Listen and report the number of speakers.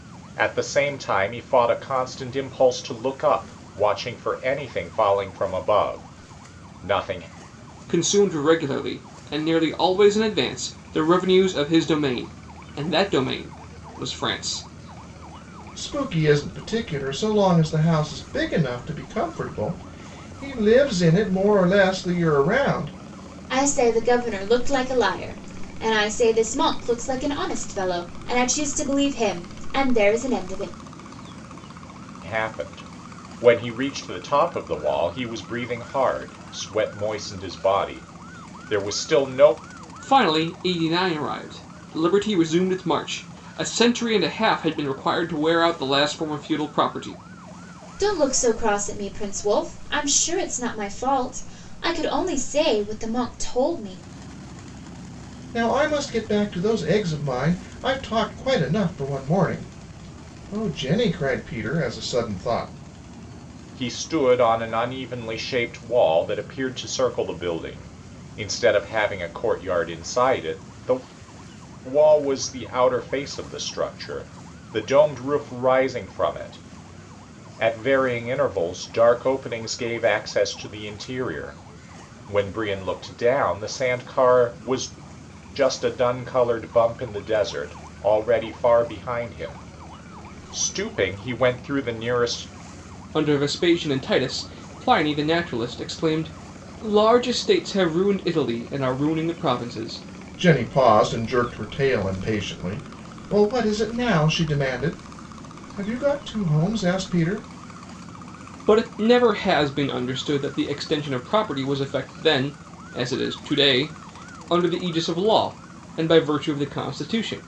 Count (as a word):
four